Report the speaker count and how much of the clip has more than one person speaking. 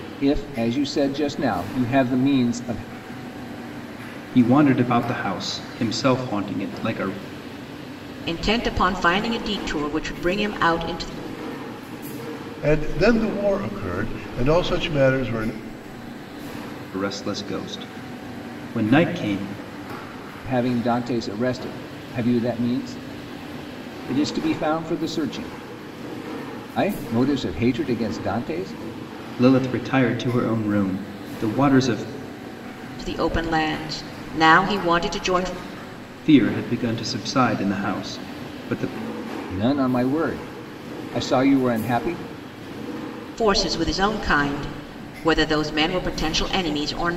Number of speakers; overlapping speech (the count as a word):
four, no overlap